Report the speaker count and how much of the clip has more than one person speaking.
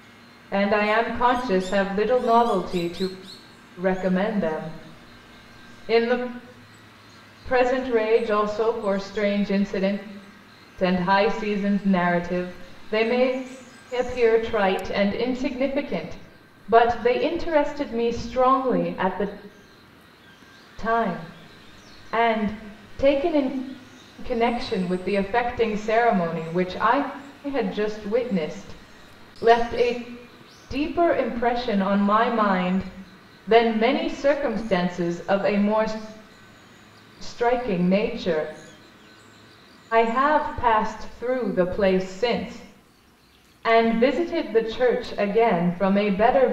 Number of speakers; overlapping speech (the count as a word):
one, no overlap